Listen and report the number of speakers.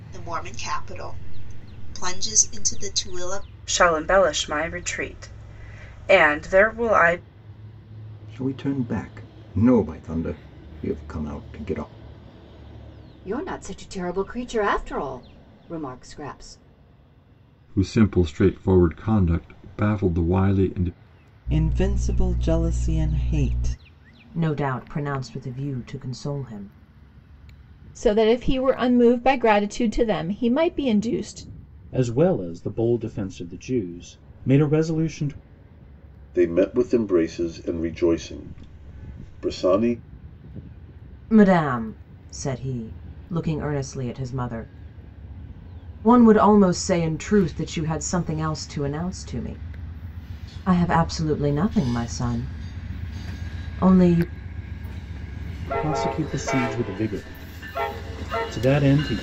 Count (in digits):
10